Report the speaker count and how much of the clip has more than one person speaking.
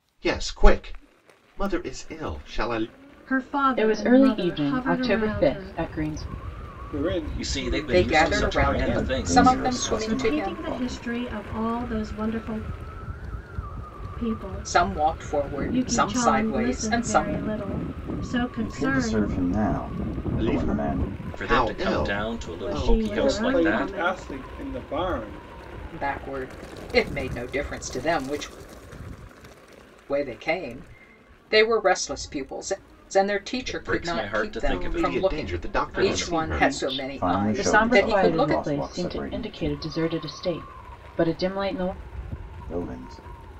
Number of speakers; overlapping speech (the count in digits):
7, about 44%